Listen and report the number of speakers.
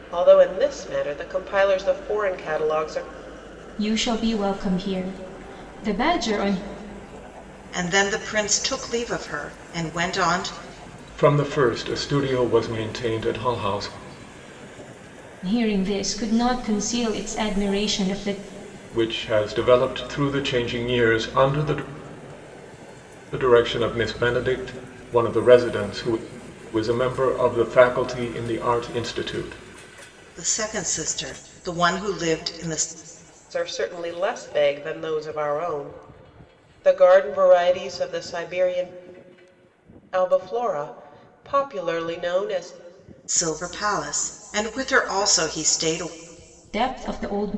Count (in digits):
4